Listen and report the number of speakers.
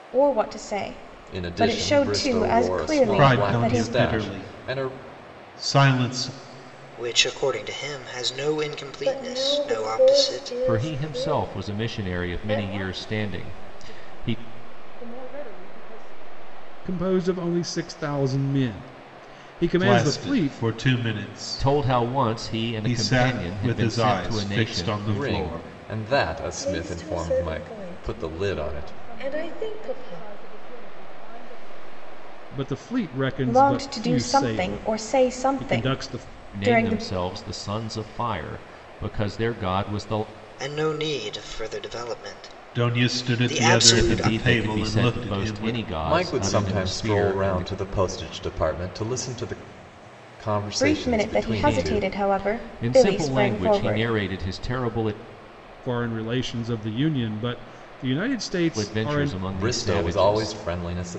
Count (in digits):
8